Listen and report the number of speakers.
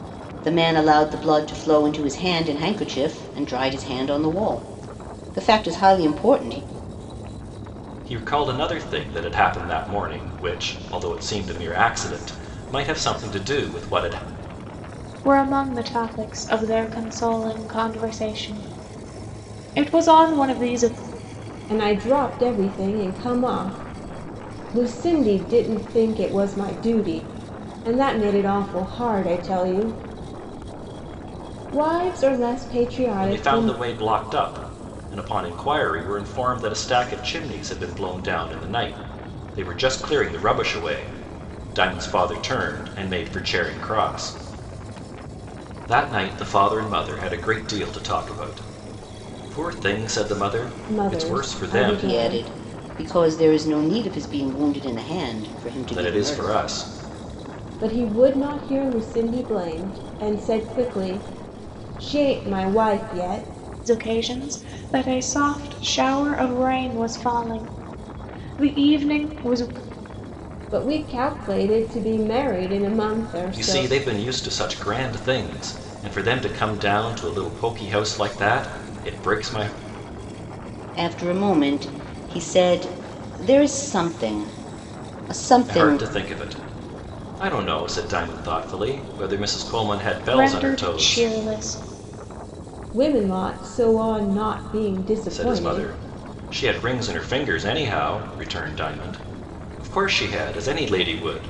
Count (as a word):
four